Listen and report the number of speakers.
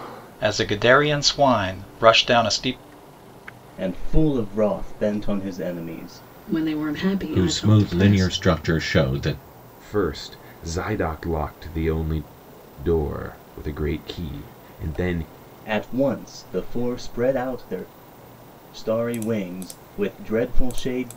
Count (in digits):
5